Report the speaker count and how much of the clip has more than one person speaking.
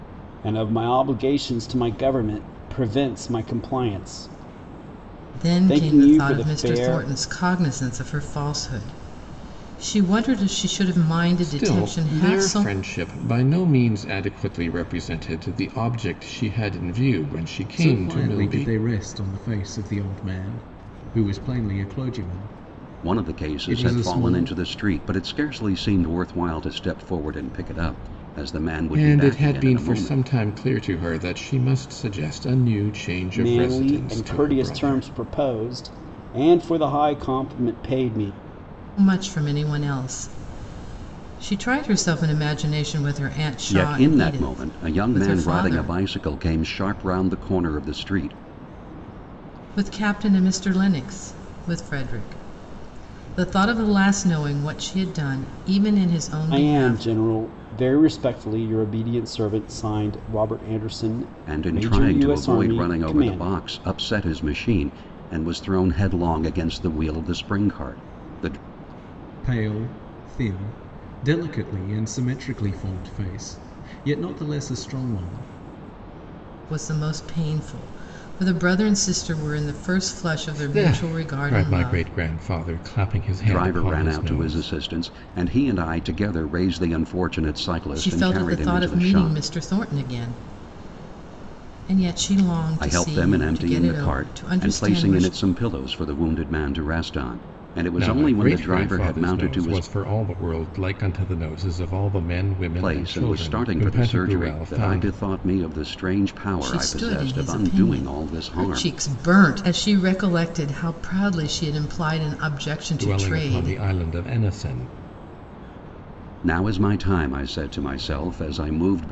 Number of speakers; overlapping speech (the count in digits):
5, about 24%